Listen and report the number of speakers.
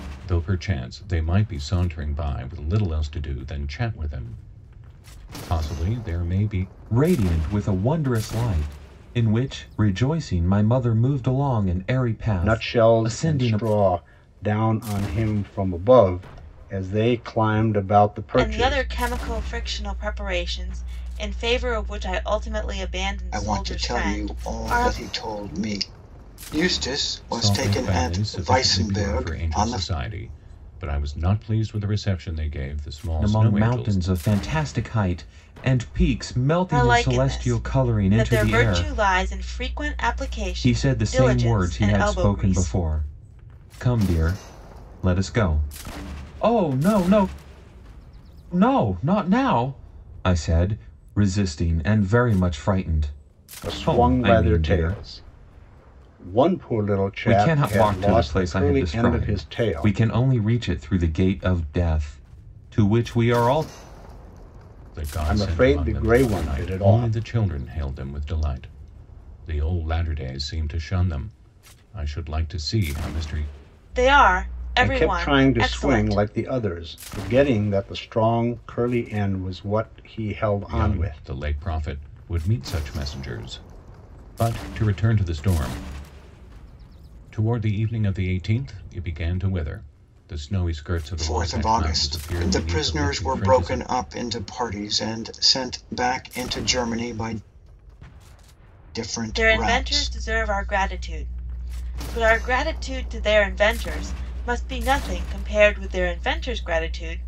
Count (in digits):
5